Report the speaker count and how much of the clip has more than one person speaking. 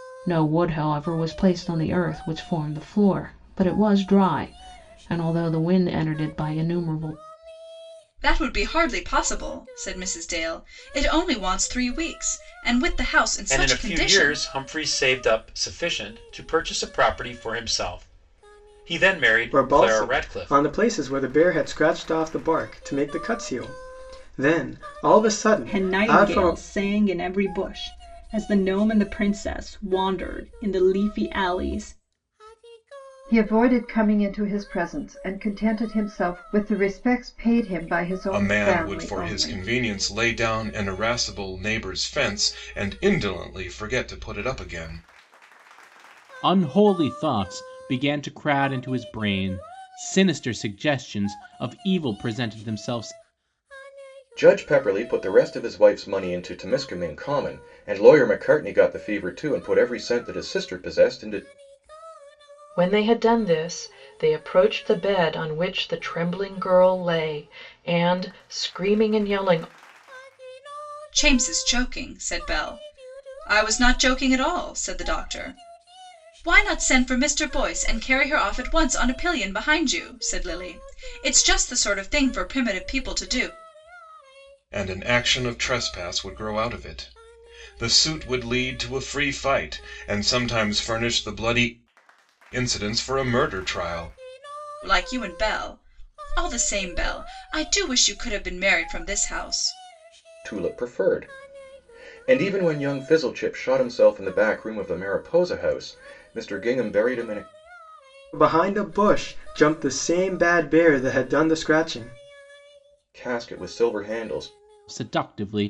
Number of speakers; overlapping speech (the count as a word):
ten, about 4%